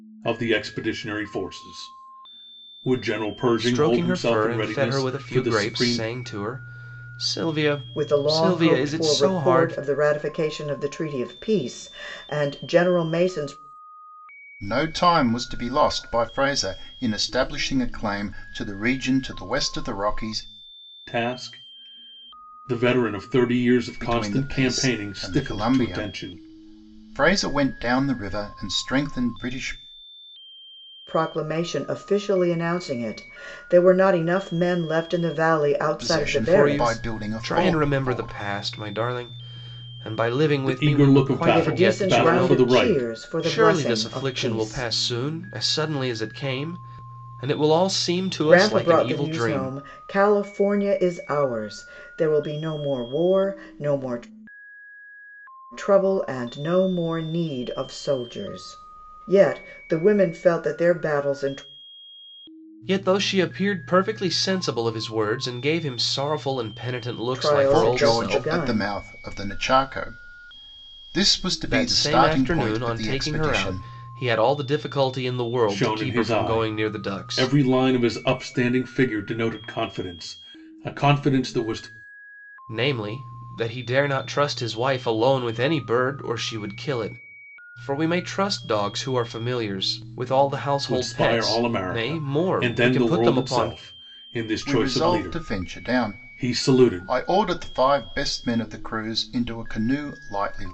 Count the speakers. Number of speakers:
4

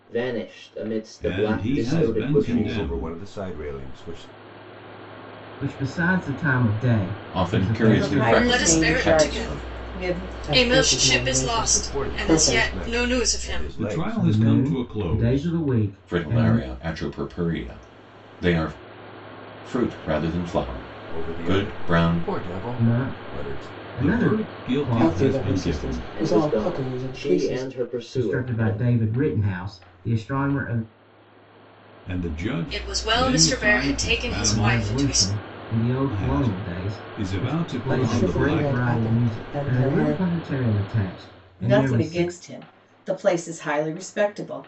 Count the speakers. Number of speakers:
8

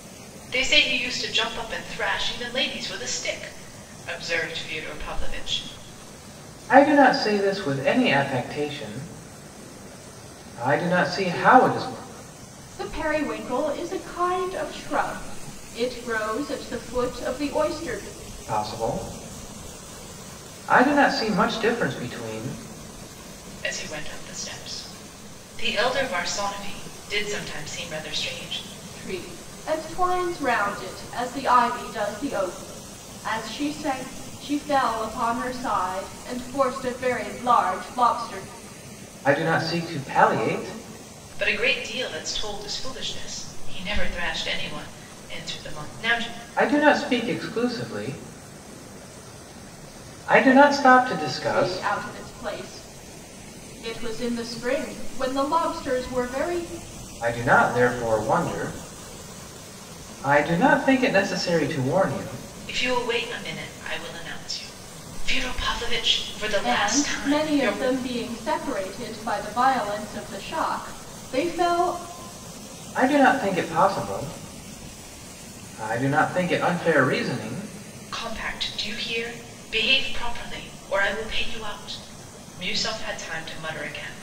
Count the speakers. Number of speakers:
3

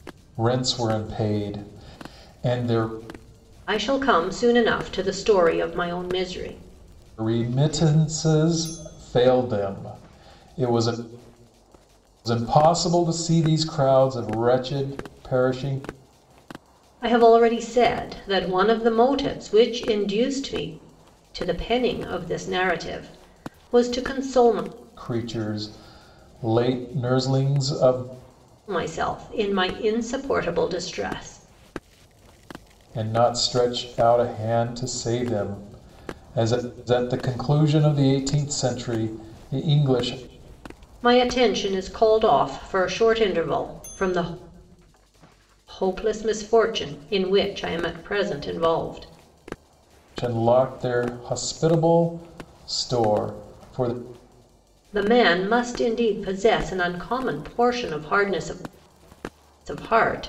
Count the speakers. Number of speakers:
2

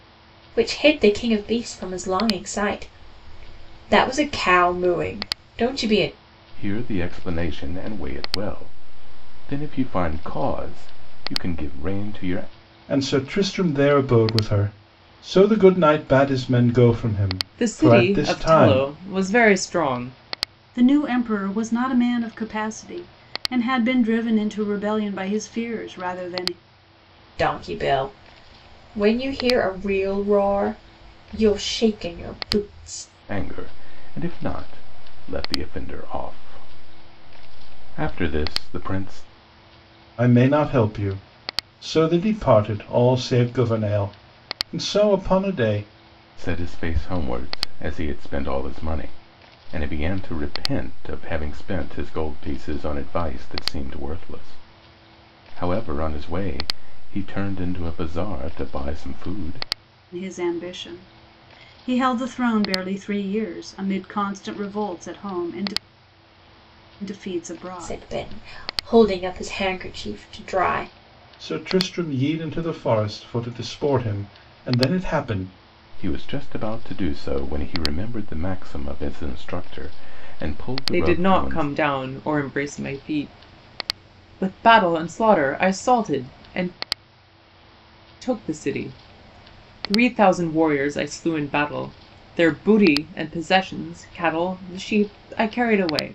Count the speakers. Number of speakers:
5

